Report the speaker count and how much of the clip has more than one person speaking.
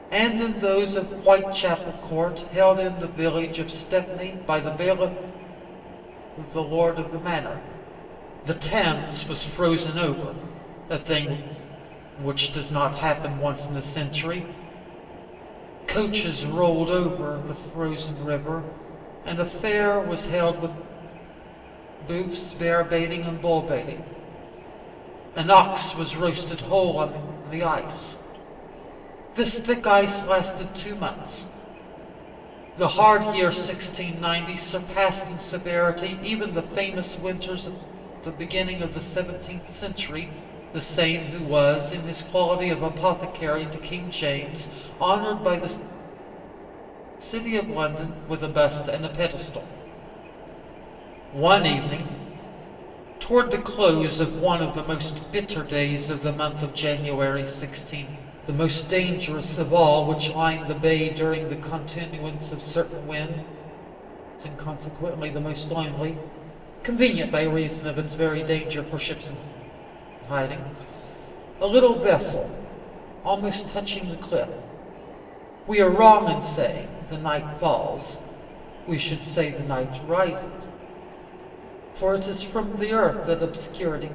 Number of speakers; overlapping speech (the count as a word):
one, no overlap